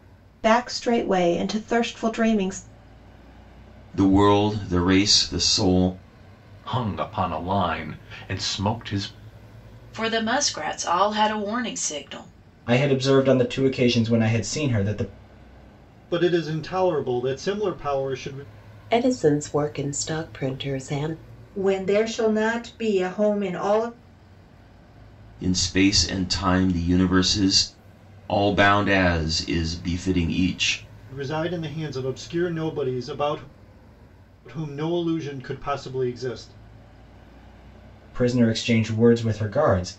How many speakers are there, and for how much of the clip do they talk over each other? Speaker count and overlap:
8, no overlap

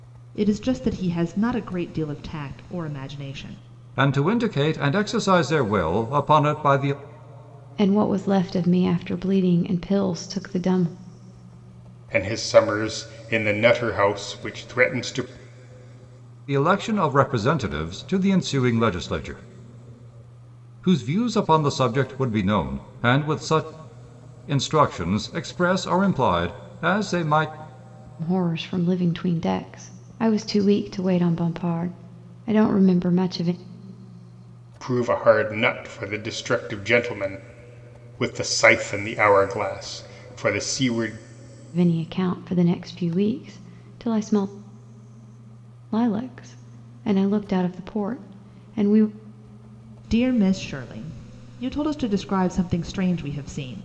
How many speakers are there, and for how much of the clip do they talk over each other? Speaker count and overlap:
4, no overlap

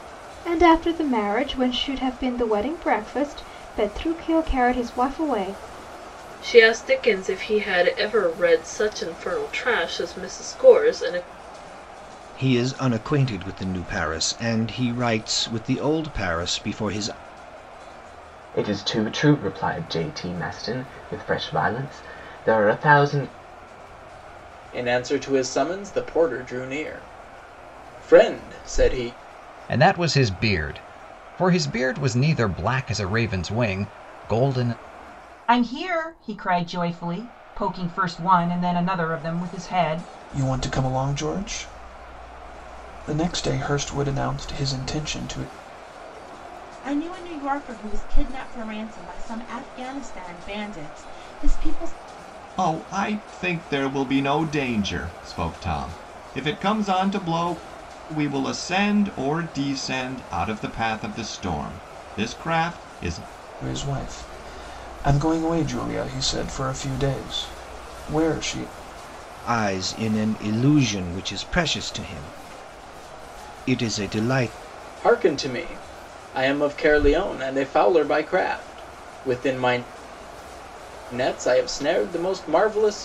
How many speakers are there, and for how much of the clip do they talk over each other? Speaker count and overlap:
10, no overlap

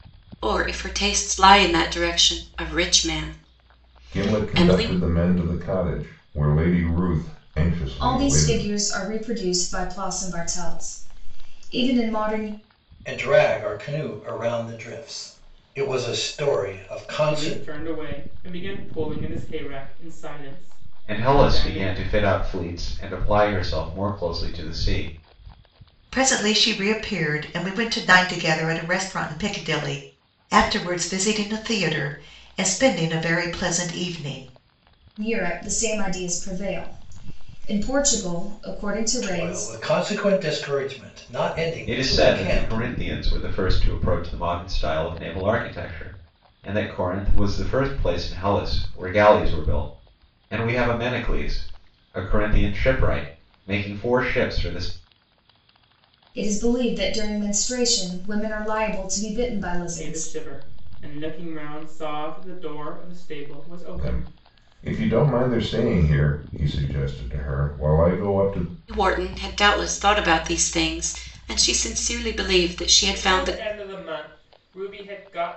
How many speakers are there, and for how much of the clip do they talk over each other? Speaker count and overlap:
7, about 8%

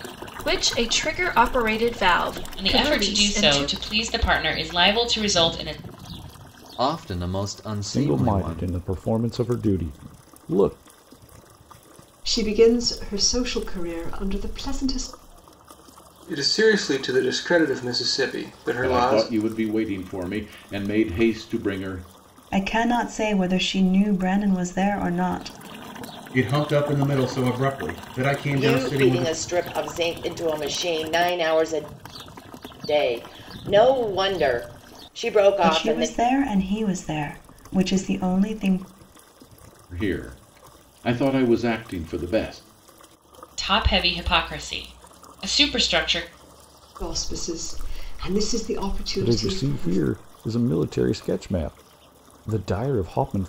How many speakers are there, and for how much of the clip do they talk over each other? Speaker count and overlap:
10, about 9%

